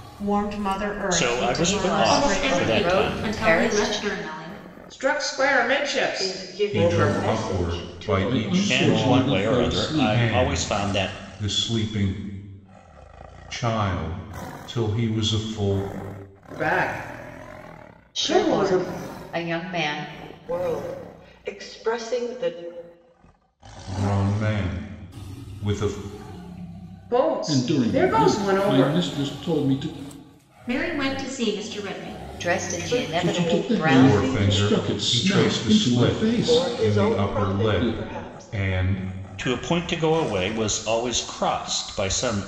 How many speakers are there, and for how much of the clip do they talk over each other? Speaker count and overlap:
eight, about 39%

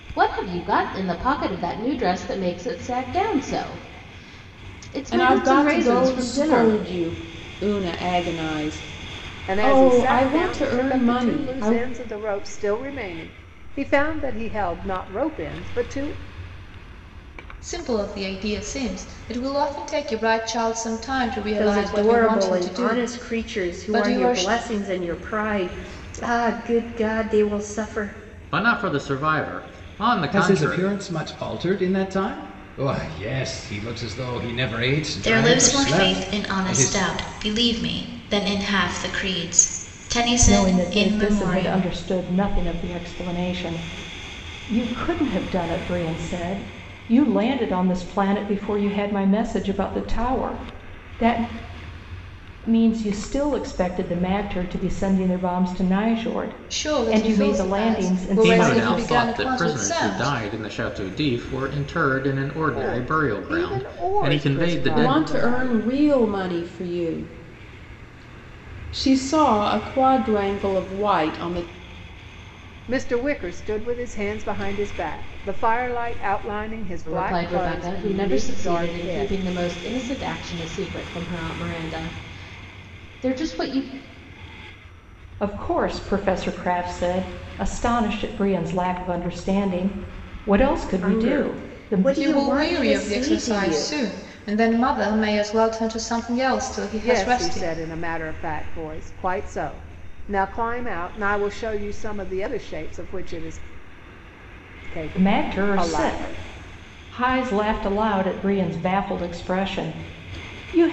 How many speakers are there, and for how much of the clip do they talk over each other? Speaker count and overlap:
nine, about 23%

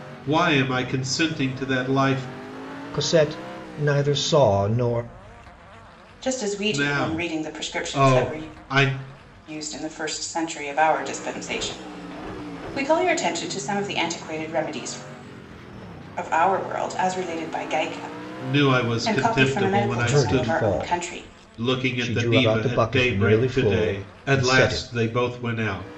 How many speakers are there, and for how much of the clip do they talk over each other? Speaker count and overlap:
three, about 28%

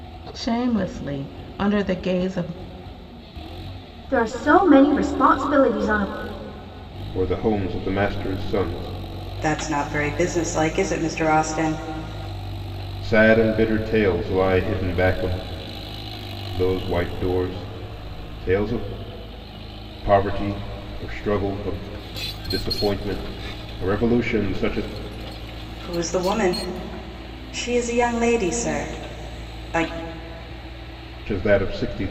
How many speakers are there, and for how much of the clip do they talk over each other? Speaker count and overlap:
four, no overlap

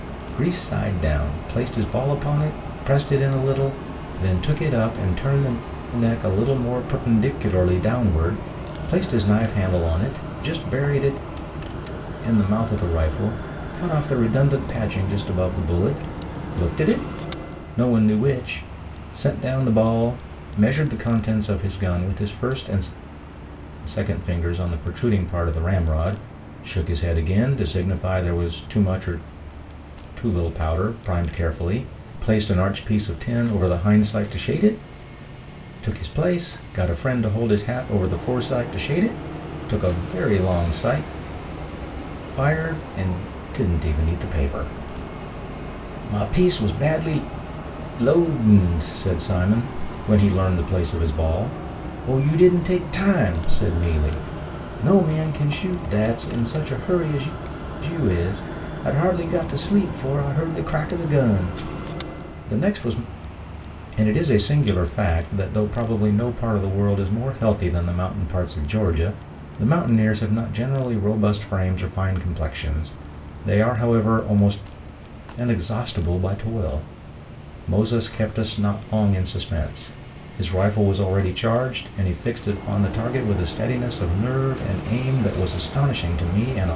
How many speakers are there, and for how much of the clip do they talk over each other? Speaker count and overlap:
one, no overlap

